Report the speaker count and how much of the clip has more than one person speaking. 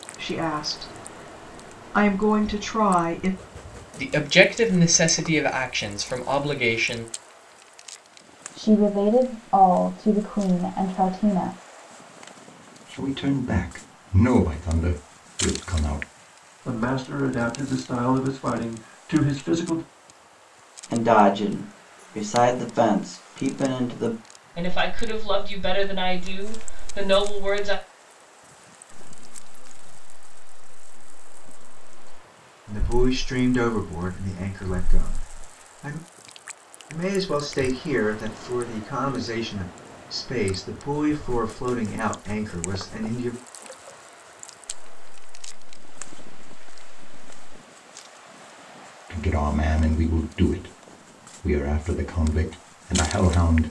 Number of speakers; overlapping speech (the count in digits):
9, no overlap